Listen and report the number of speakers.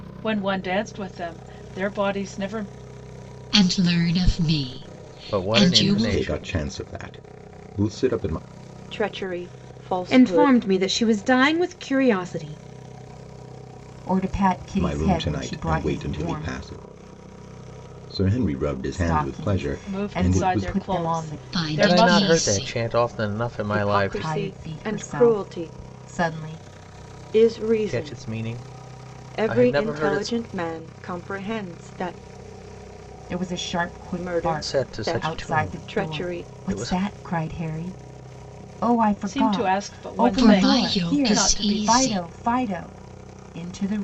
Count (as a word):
seven